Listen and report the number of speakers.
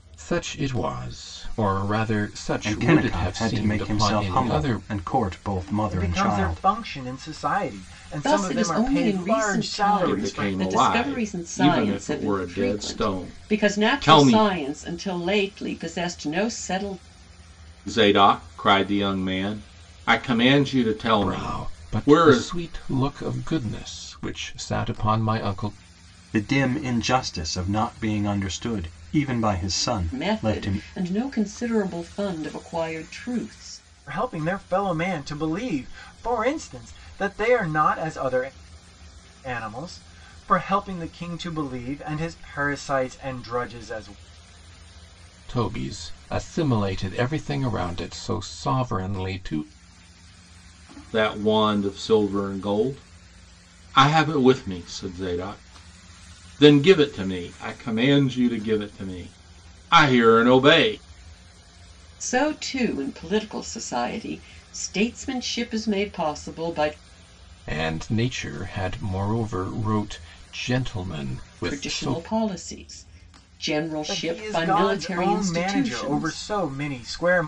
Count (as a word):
five